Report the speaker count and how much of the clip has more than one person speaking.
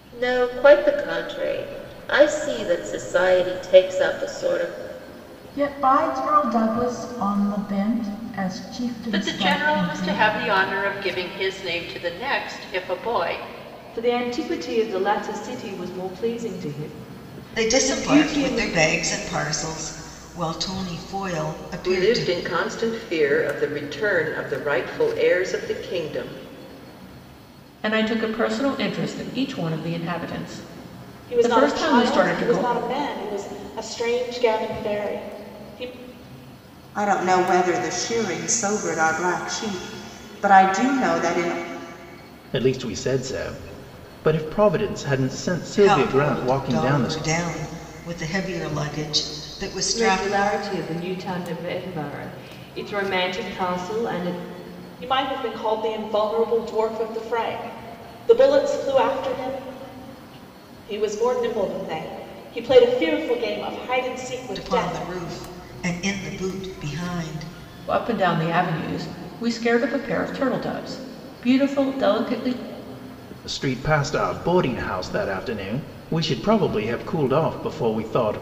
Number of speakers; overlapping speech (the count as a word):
ten, about 9%